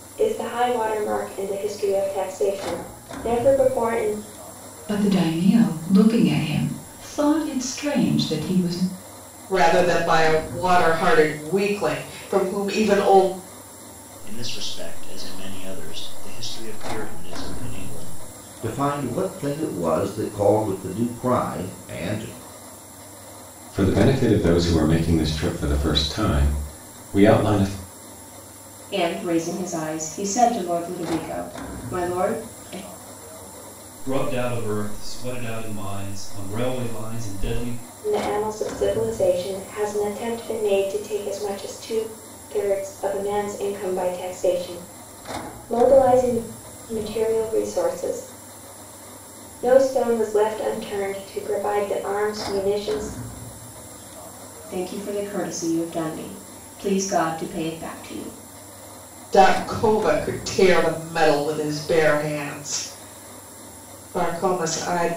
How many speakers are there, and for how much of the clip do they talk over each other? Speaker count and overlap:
eight, no overlap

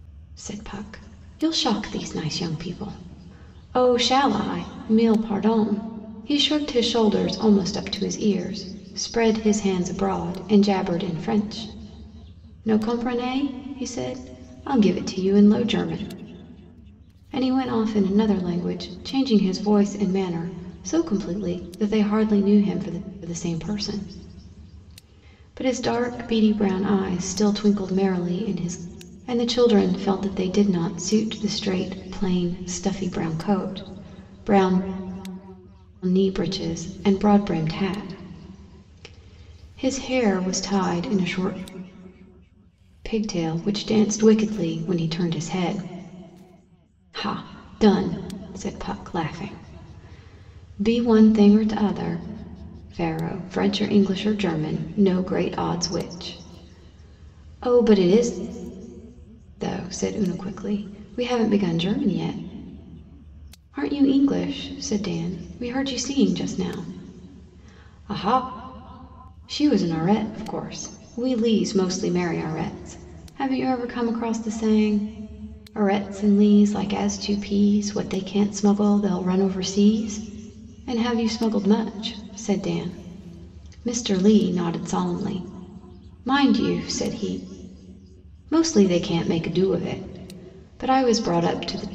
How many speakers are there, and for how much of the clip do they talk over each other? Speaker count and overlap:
one, no overlap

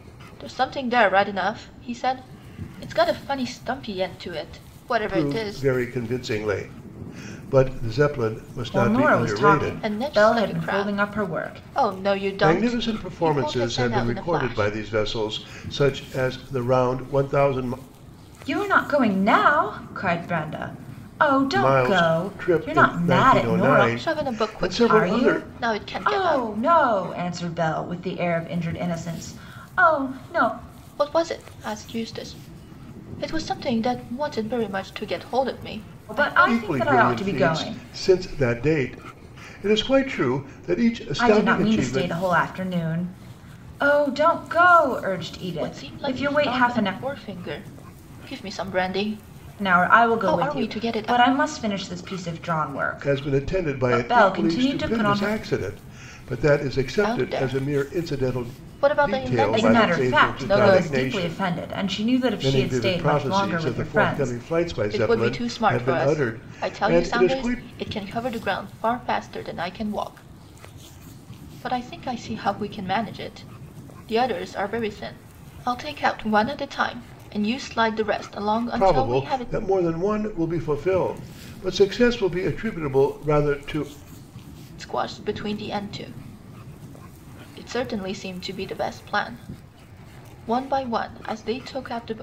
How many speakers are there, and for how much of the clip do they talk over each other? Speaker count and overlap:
three, about 31%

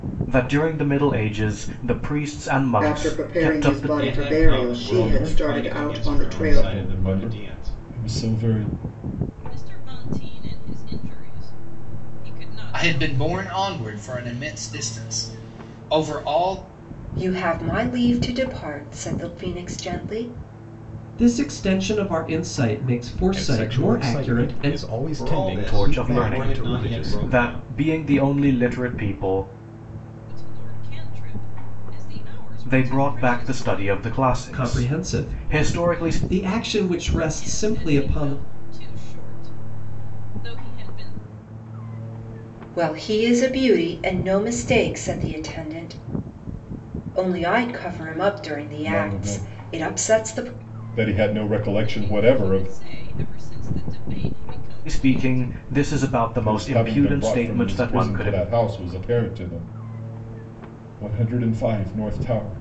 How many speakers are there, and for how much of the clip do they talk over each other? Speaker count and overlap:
nine, about 31%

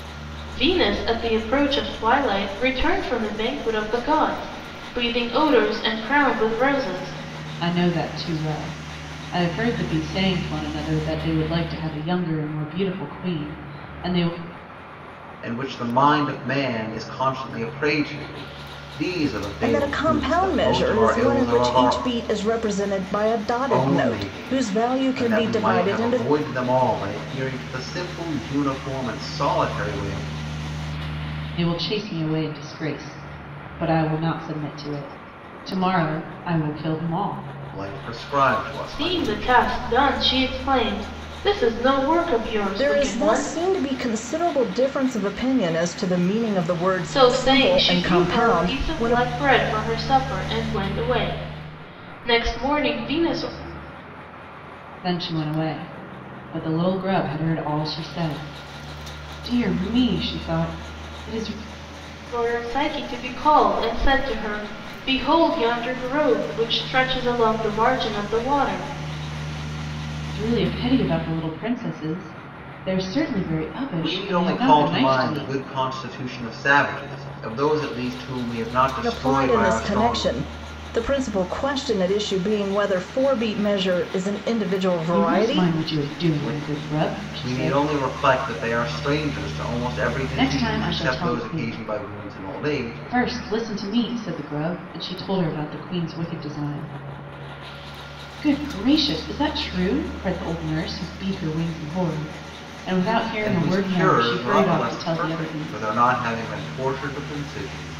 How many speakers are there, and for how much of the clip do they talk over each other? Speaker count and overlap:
four, about 18%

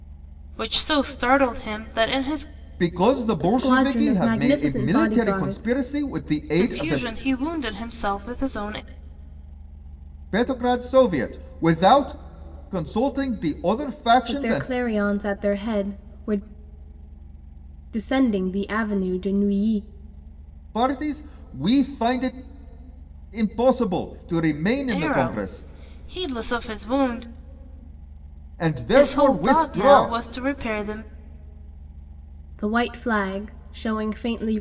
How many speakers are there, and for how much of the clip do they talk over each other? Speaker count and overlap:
three, about 16%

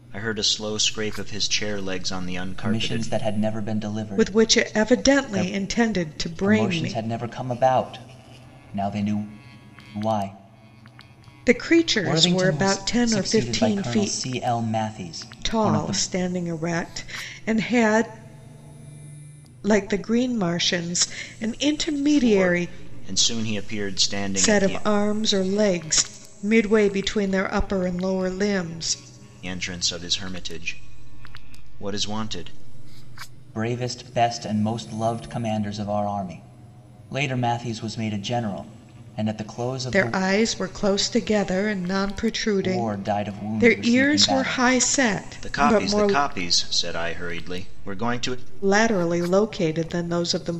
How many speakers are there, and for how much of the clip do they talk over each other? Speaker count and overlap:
three, about 19%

